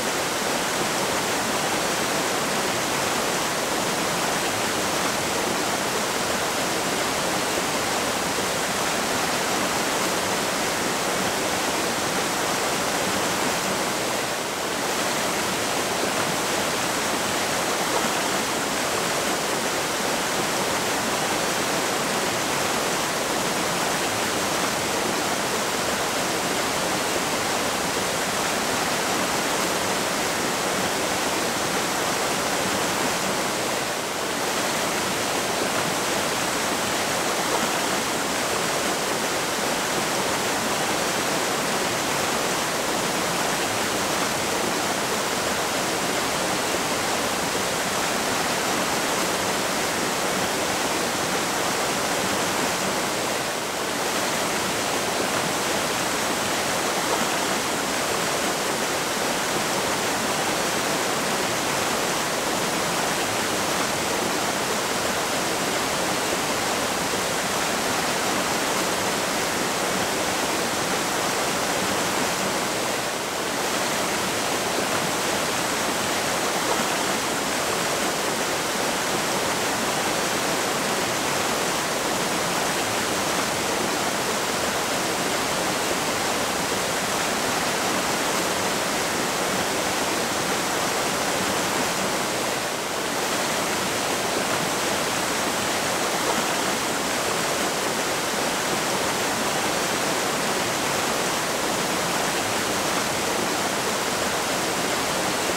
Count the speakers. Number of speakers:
zero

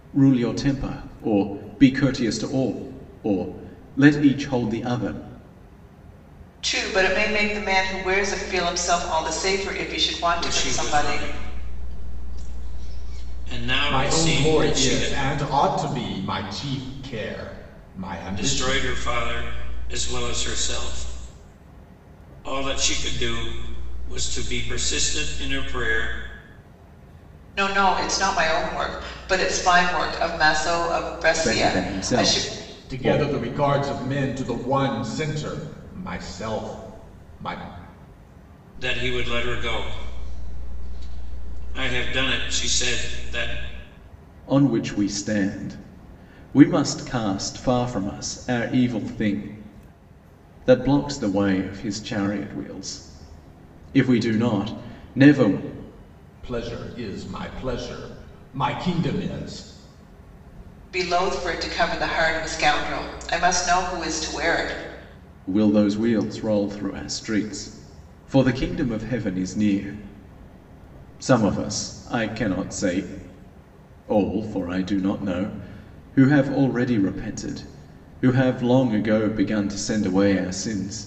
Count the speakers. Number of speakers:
four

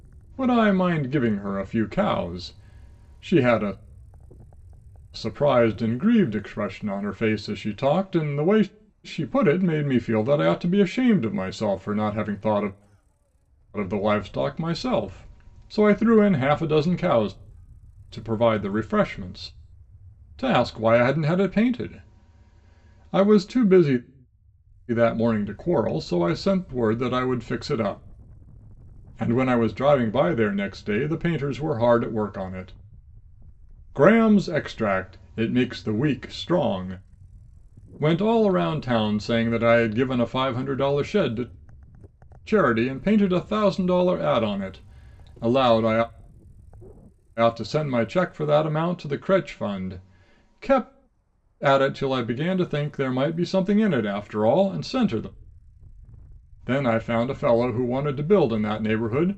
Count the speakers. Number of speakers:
one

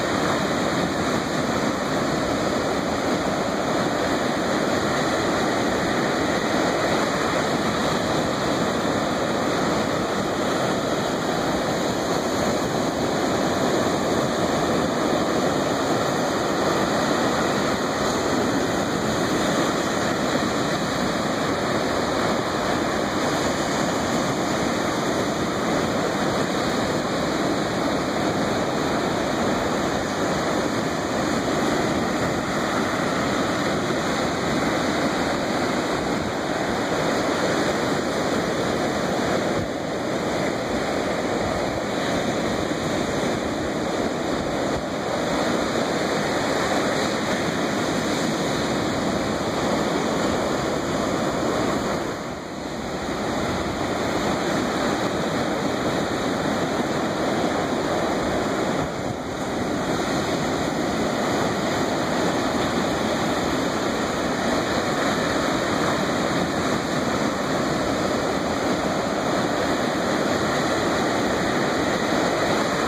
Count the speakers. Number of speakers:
zero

